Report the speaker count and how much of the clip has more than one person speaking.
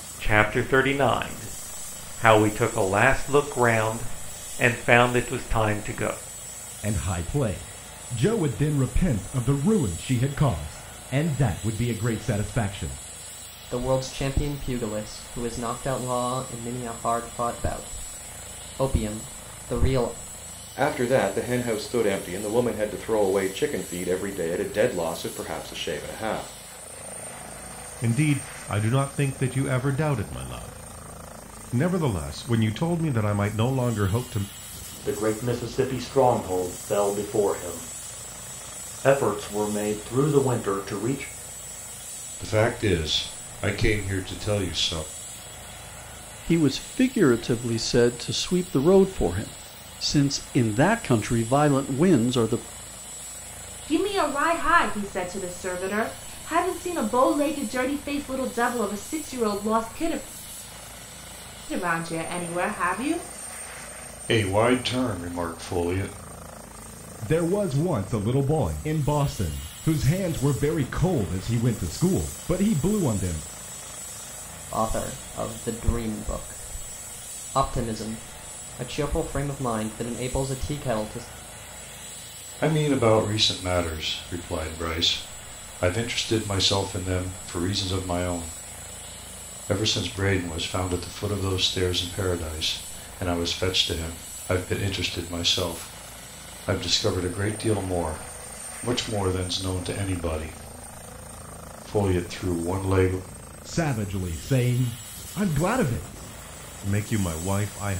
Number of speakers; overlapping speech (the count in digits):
9, no overlap